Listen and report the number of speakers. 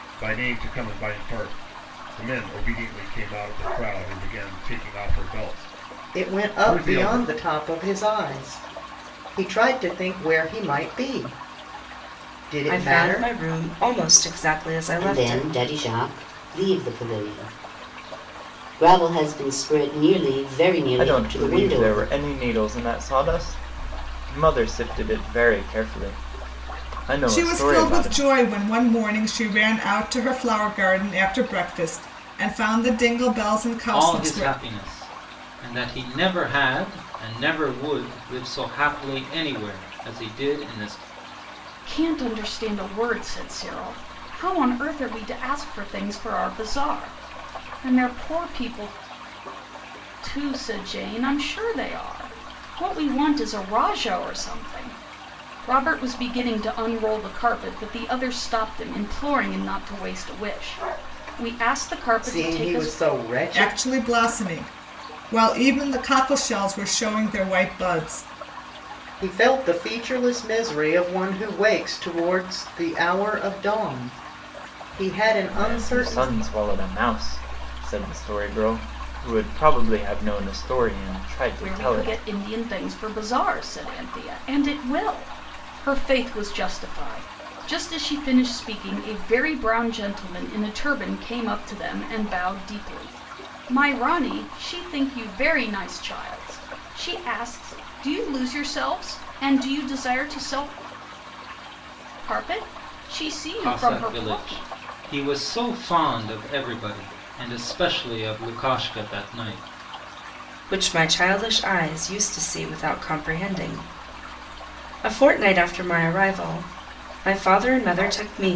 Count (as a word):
eight